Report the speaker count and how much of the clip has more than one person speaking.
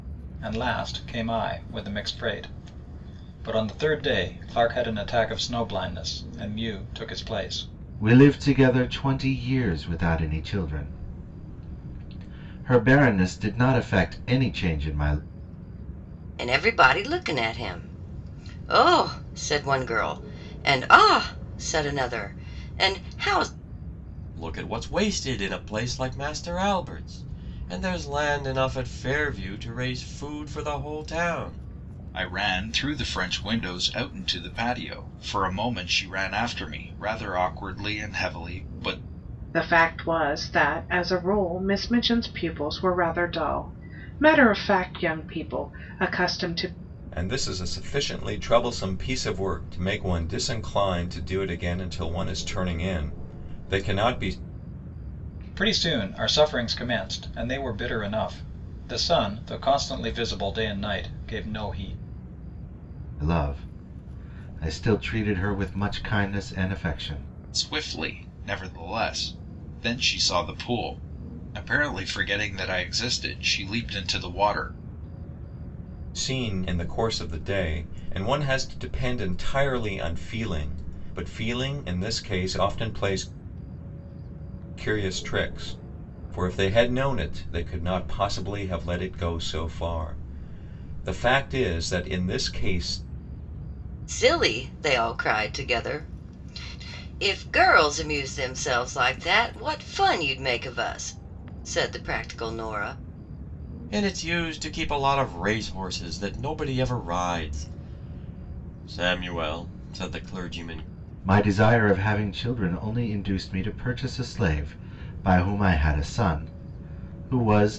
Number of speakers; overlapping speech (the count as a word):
seven, no overlap